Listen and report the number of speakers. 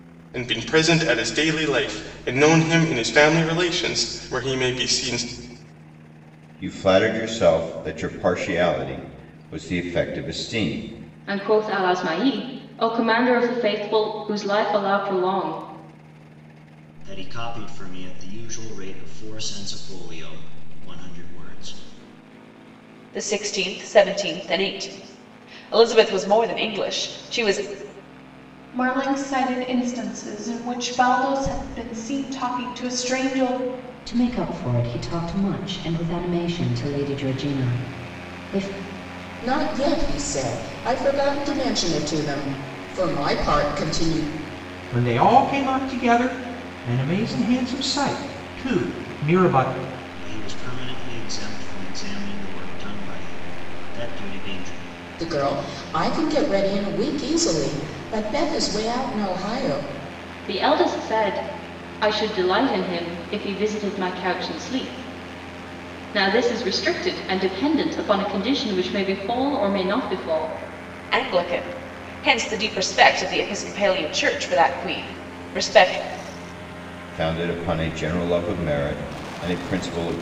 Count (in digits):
9